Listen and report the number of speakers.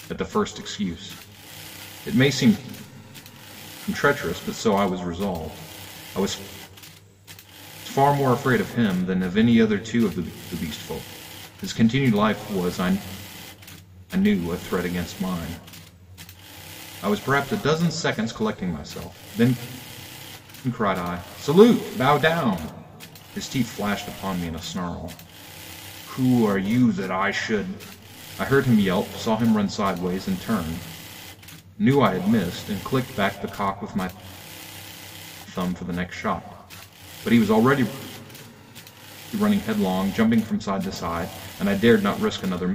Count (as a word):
one